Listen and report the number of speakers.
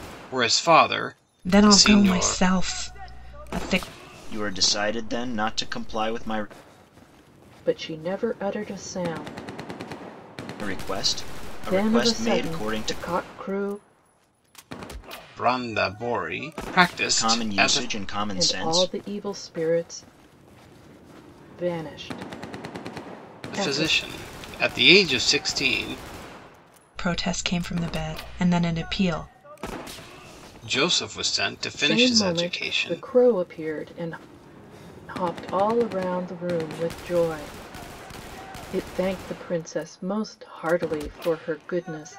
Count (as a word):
four